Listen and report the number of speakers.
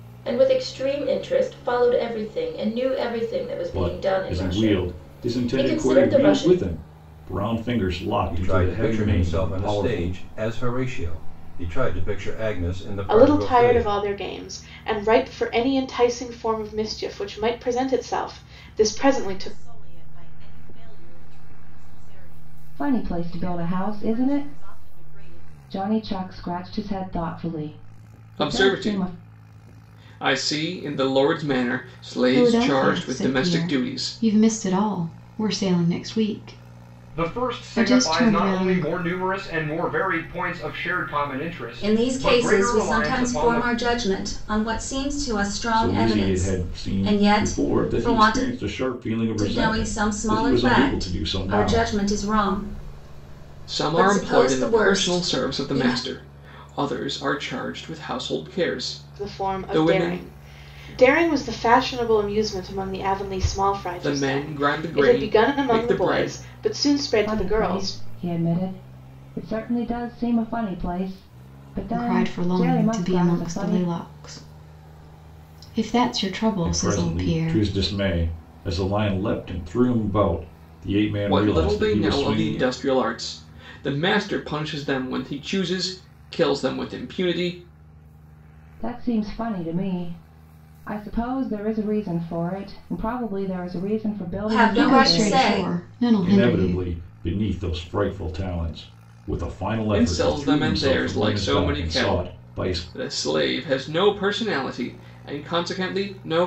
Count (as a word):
ten